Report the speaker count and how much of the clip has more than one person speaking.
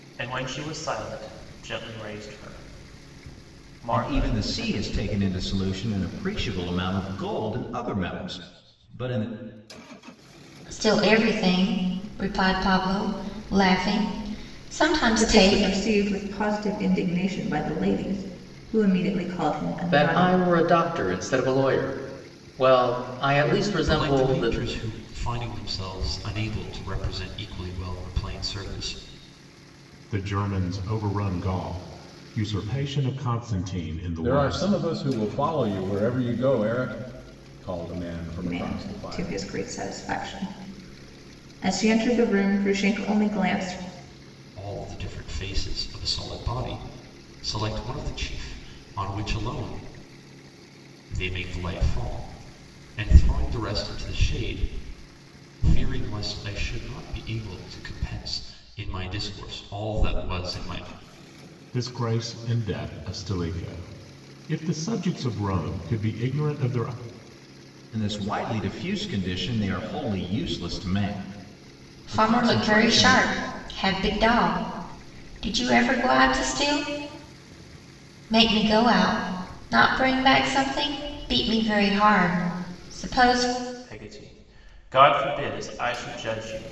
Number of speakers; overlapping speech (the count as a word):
eight, about 7%